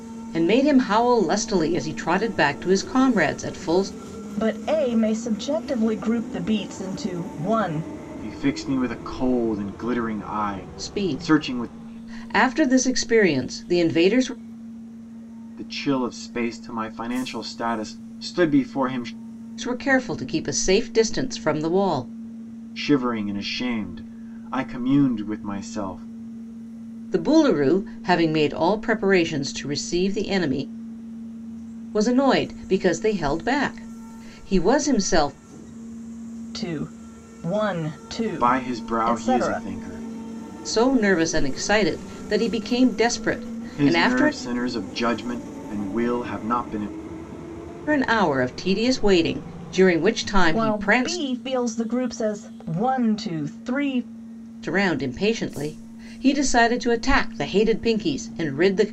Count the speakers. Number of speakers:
three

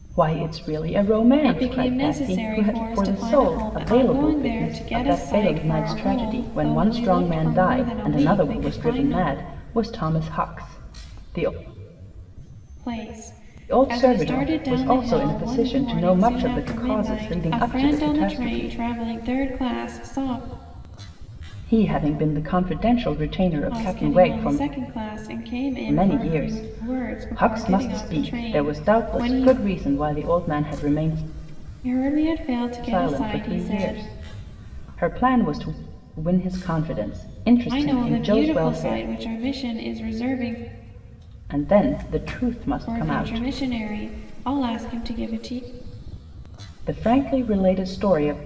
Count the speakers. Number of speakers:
two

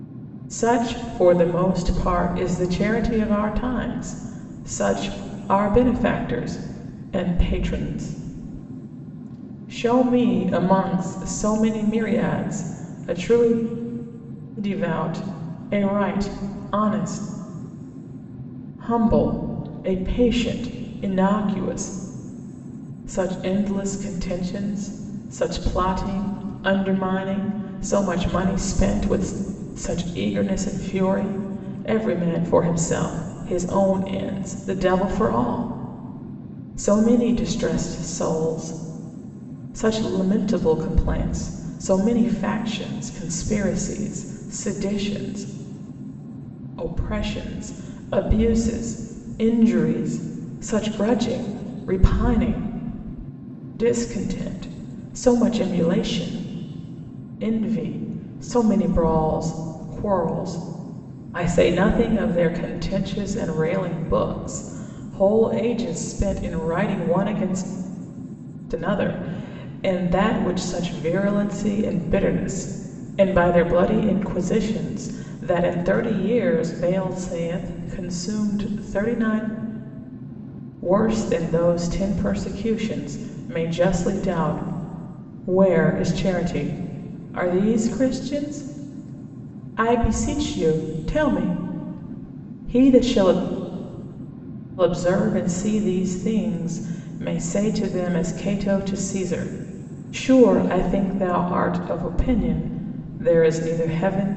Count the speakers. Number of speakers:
one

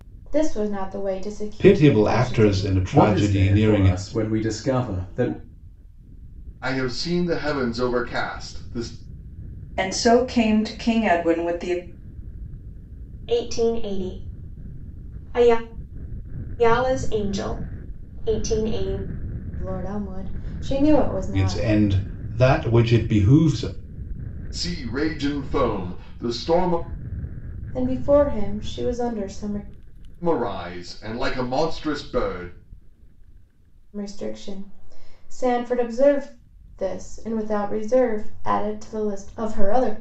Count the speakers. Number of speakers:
six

